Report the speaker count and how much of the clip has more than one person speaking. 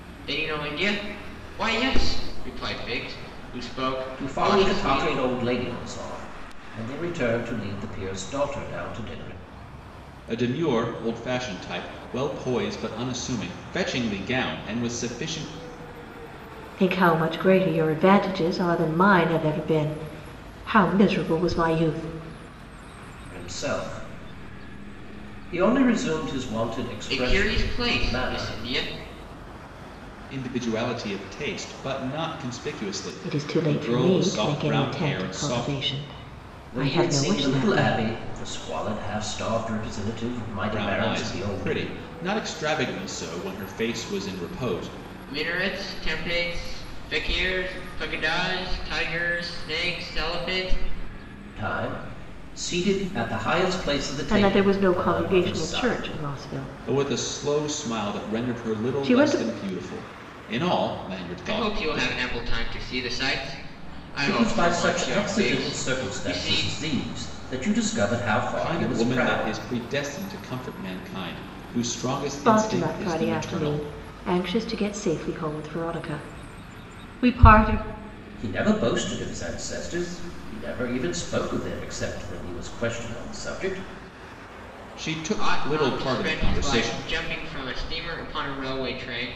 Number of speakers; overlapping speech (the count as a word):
four, about 22%